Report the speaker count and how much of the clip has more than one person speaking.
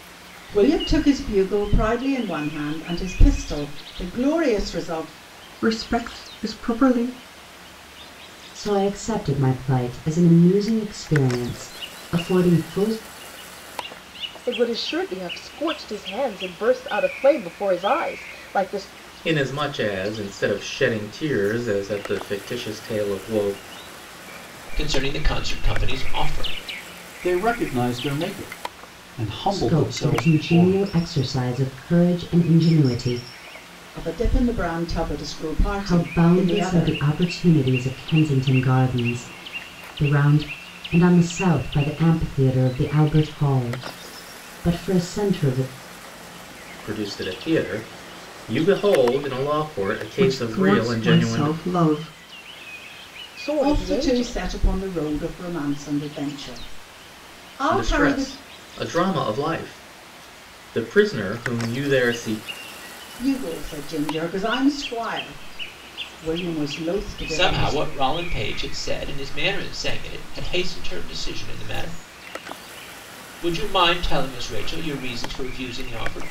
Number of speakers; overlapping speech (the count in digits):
7, about 8%